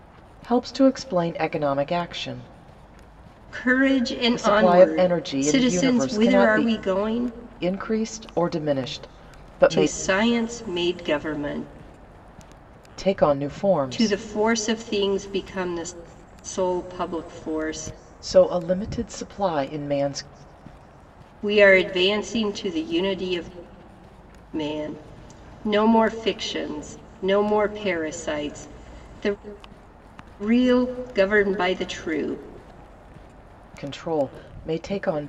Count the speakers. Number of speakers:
2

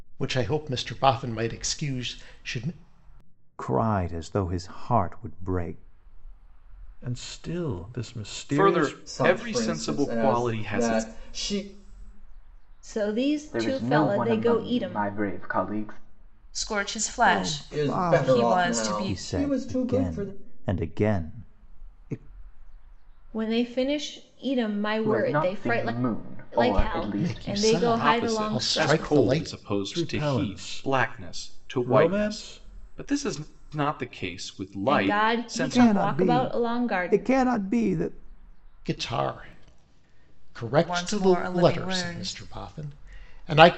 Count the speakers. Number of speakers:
8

